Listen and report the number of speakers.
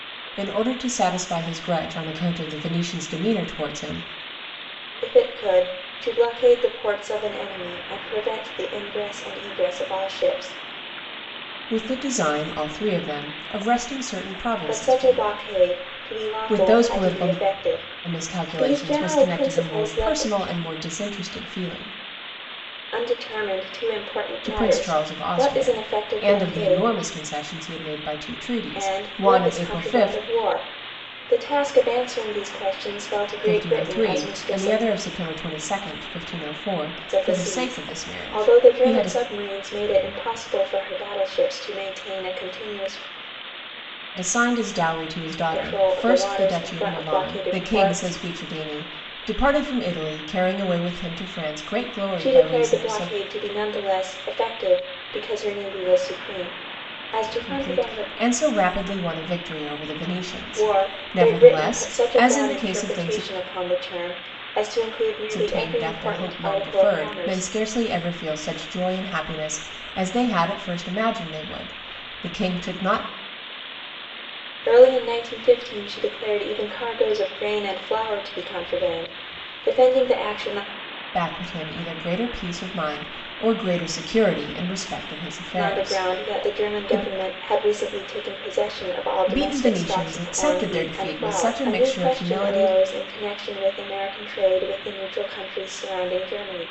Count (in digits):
2